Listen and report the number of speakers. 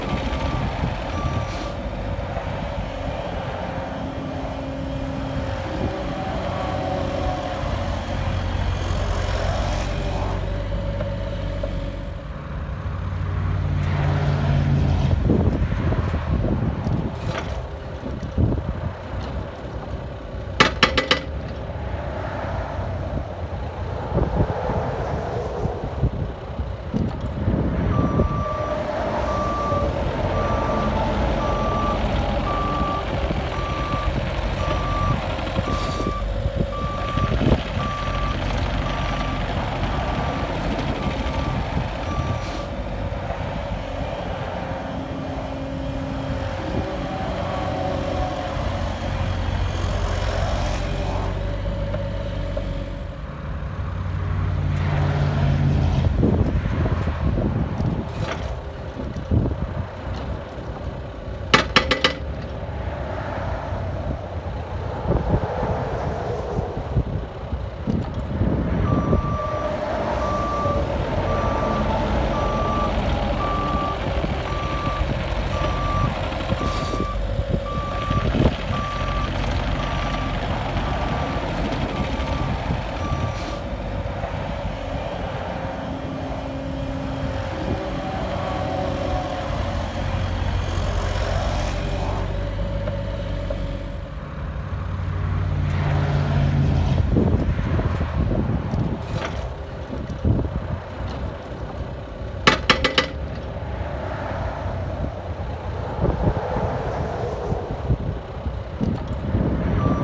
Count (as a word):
zero